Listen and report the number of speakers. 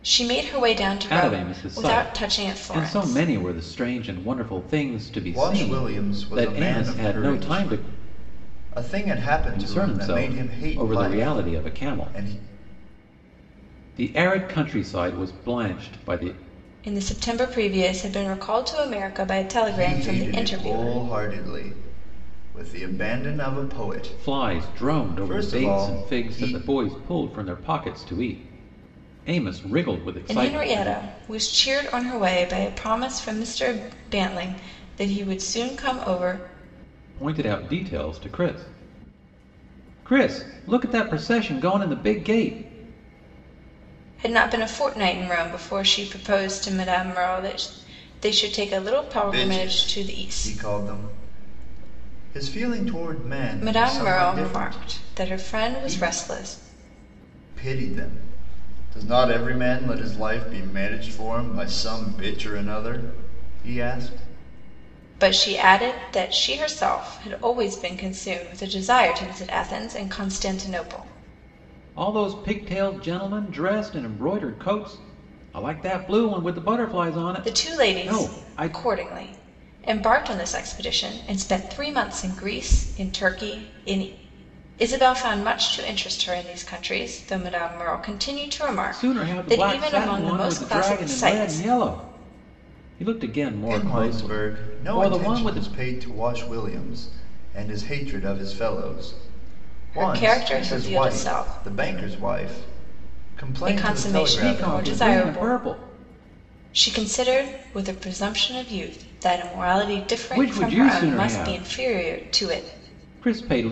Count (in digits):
3